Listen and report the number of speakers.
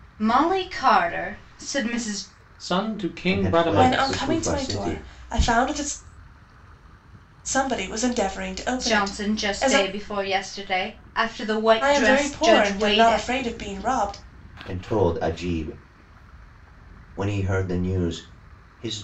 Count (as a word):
four